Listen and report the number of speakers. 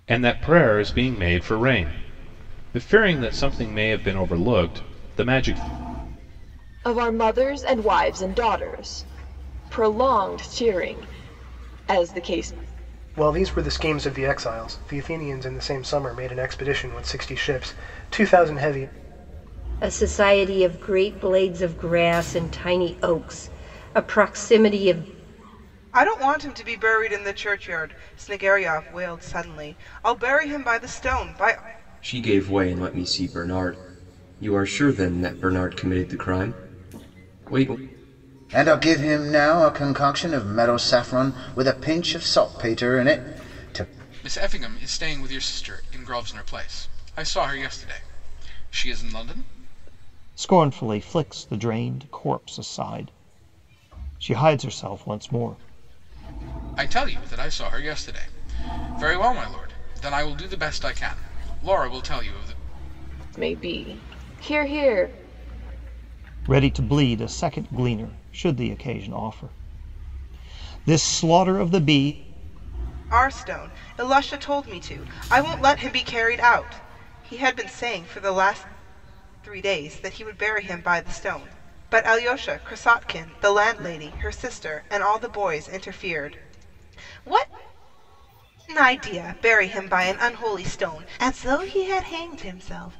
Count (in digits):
9